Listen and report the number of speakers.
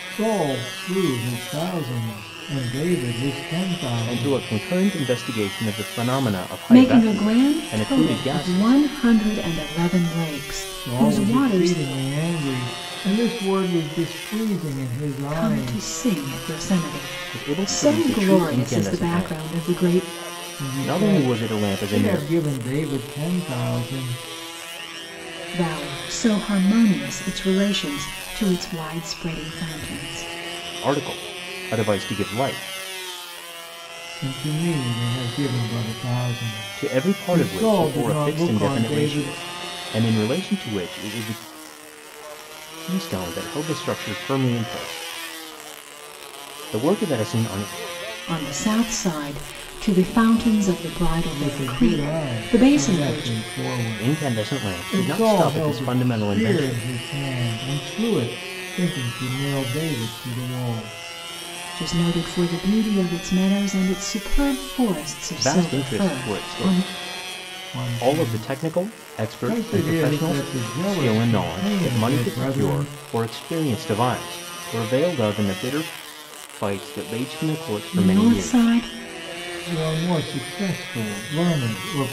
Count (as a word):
three